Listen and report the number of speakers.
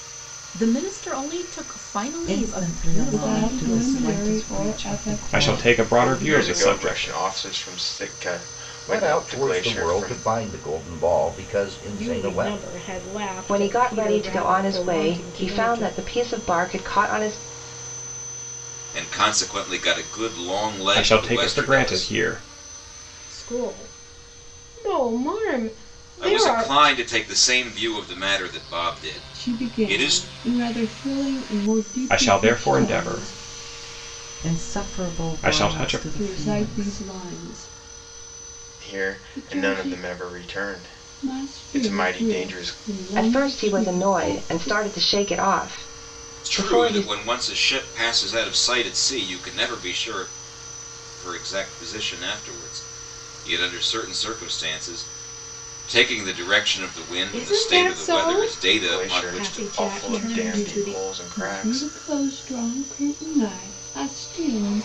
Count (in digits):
9